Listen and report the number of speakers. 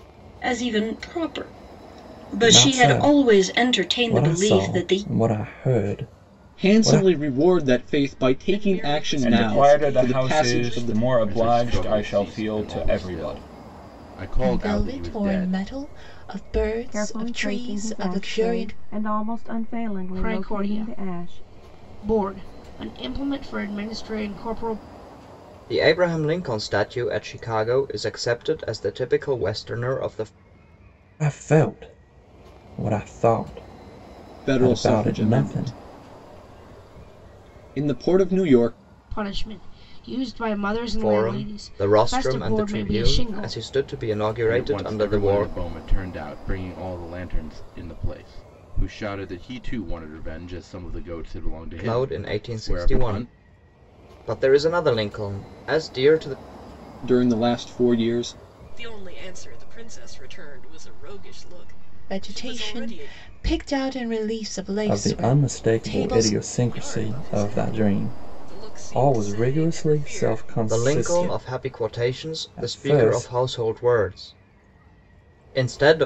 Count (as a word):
ten